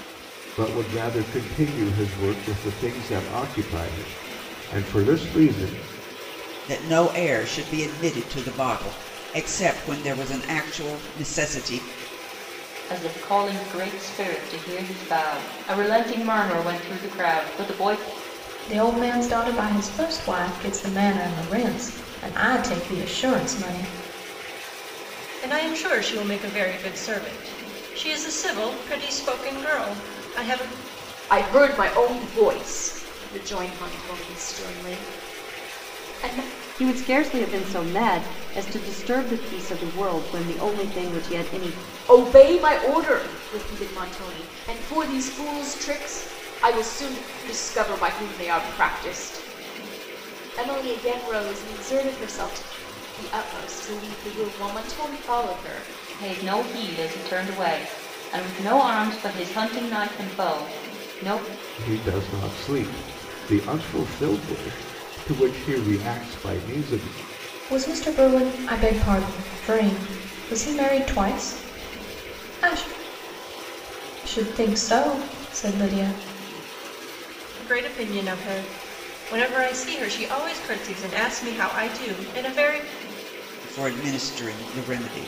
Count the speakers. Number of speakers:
seven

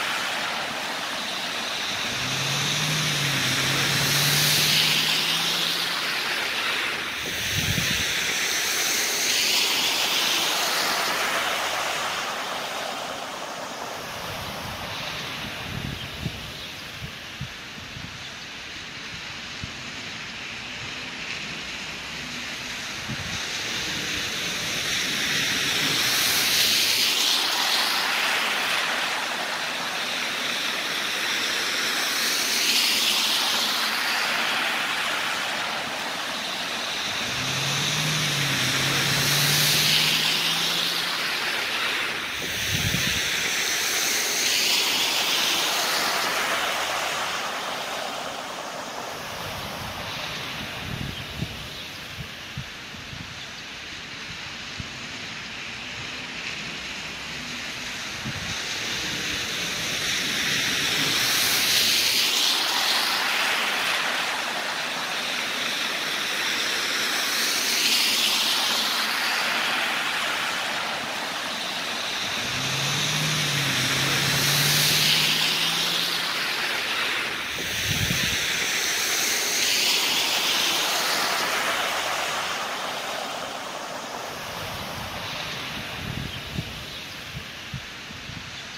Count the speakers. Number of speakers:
zero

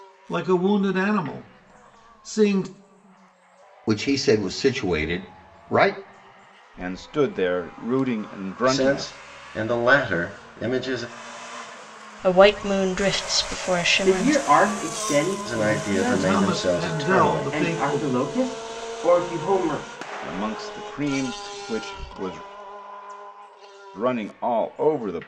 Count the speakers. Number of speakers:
six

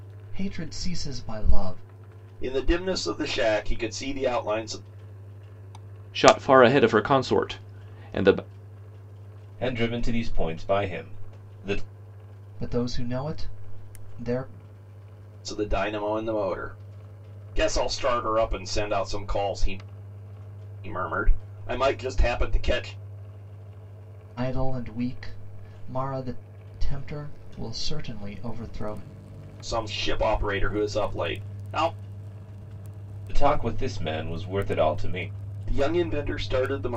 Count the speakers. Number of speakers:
four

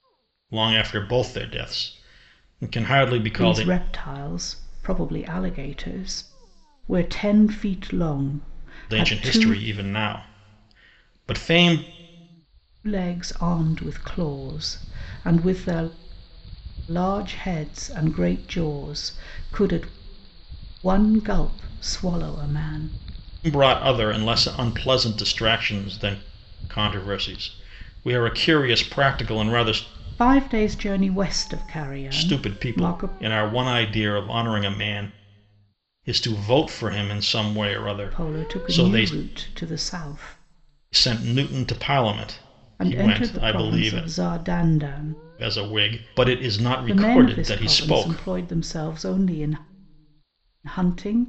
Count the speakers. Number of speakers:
two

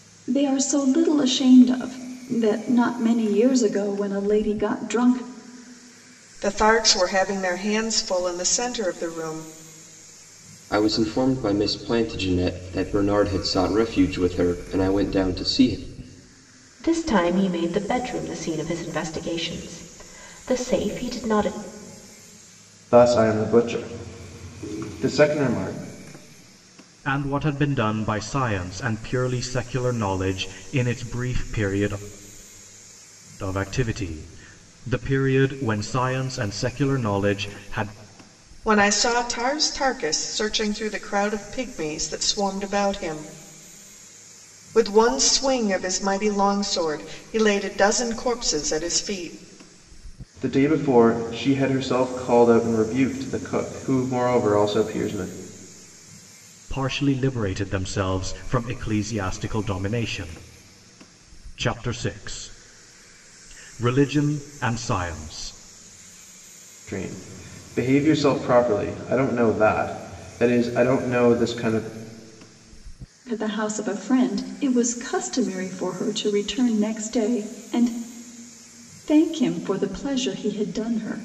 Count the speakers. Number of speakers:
six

